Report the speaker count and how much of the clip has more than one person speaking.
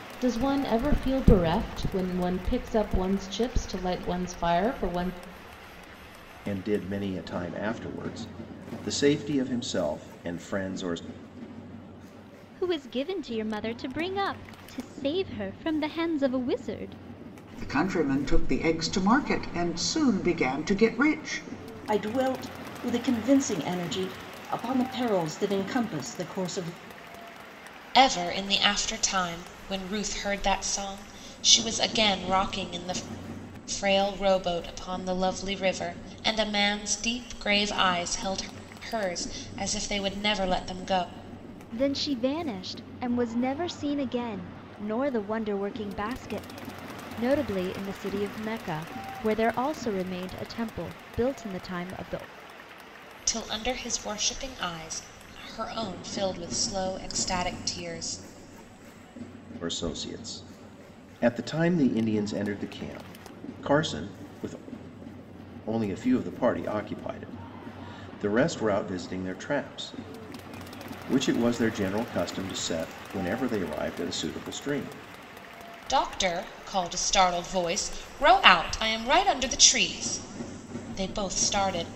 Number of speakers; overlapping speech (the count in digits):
6, no overlap